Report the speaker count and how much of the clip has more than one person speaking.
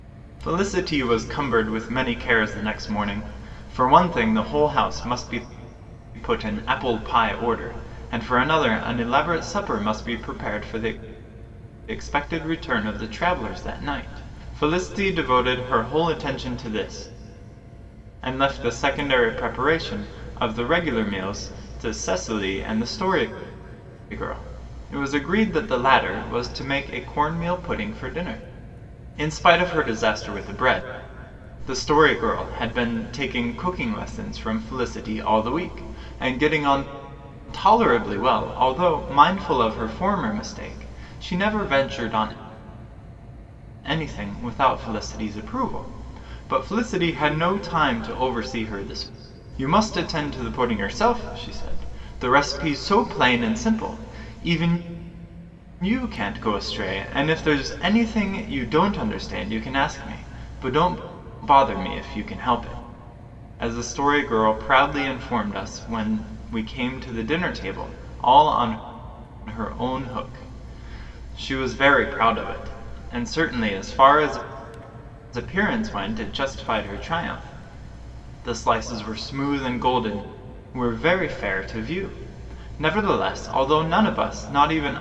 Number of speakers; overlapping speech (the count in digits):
1, no overlap